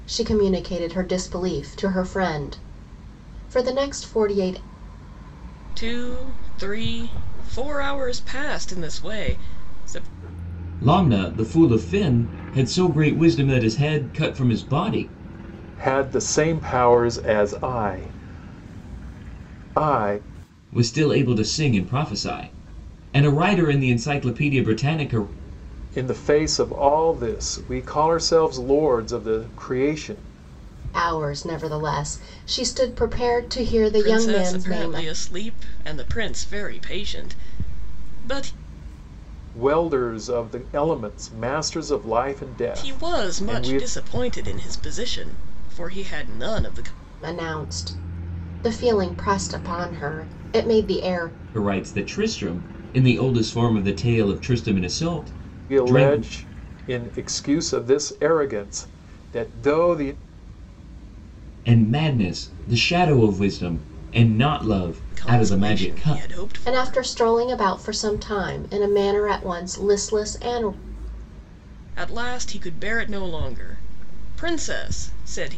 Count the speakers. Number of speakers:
four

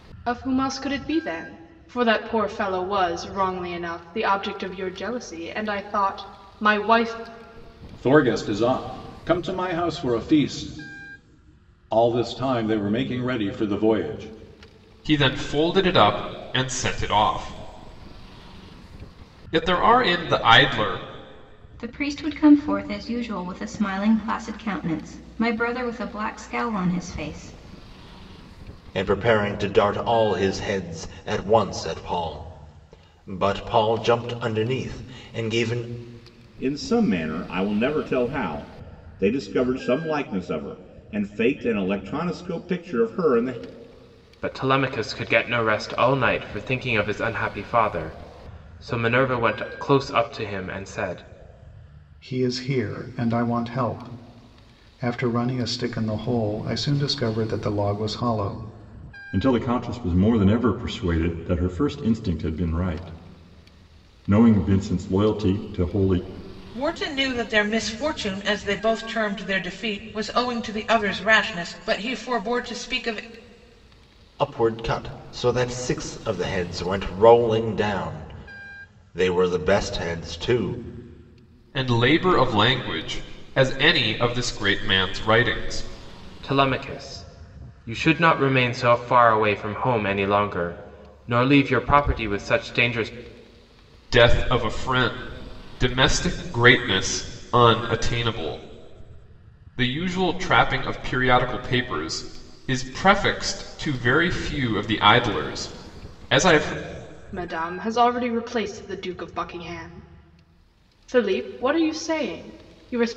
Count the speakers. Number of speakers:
ten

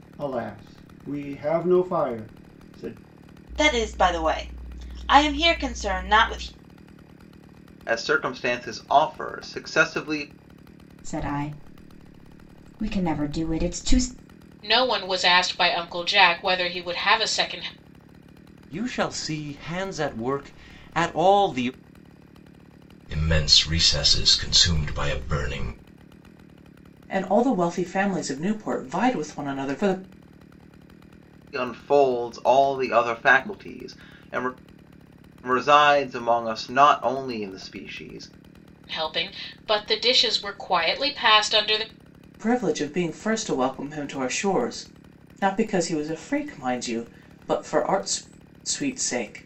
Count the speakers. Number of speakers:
eight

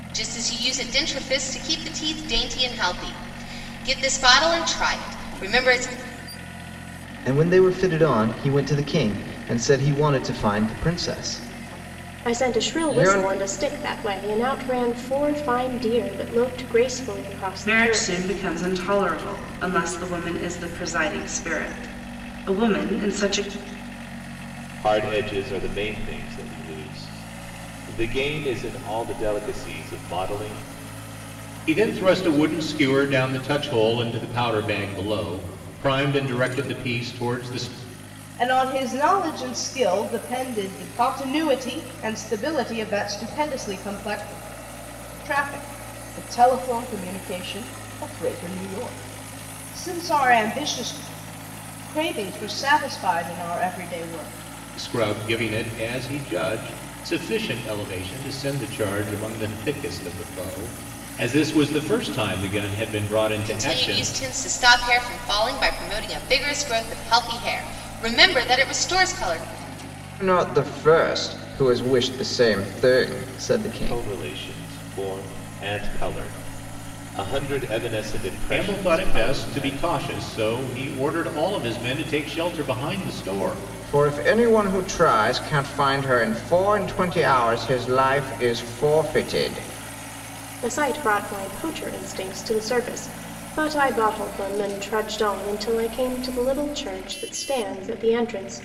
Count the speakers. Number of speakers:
seven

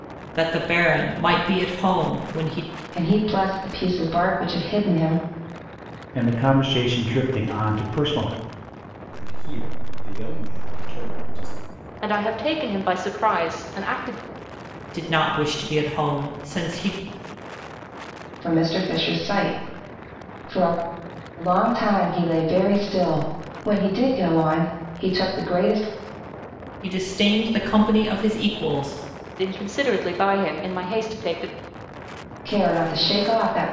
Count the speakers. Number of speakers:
five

